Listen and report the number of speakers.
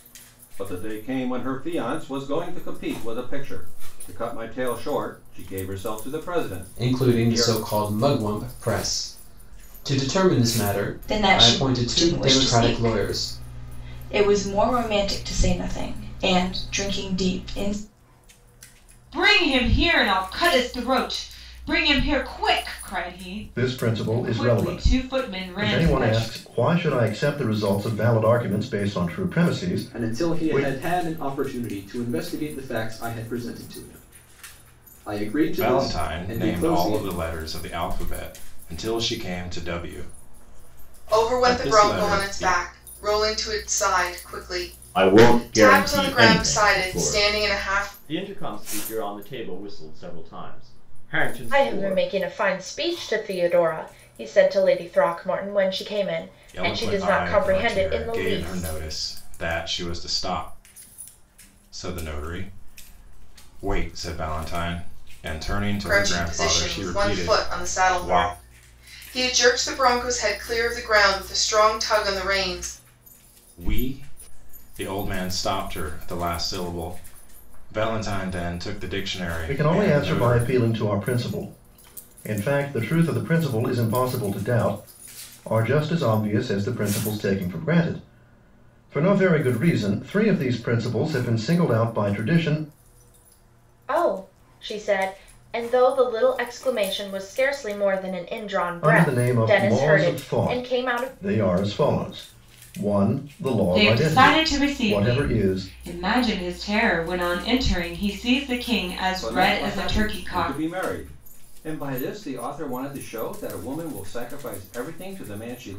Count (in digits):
10